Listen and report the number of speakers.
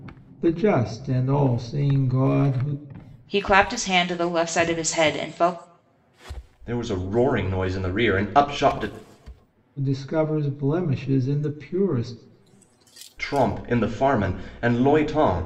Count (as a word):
three